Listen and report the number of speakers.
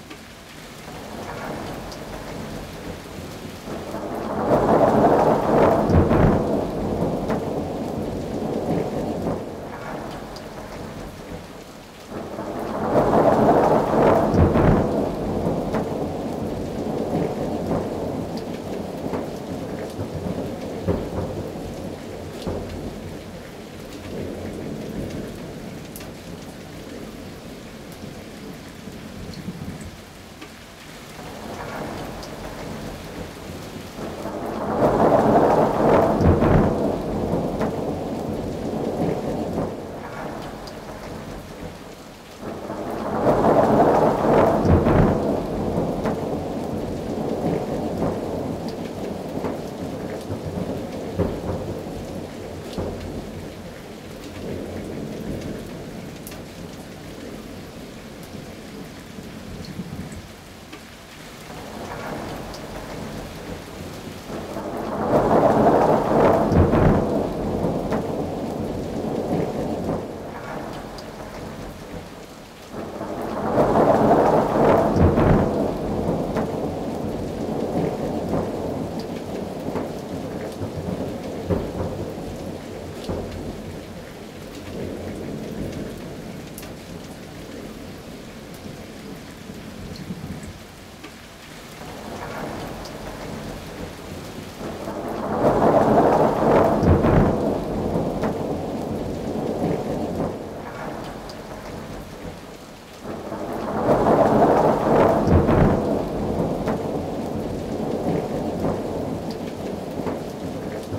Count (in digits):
0